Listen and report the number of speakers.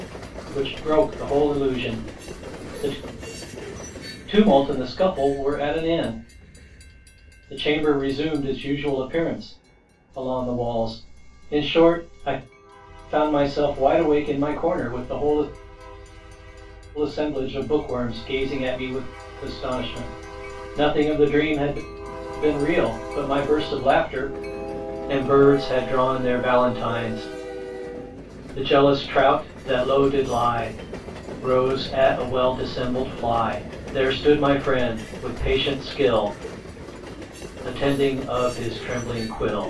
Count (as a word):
one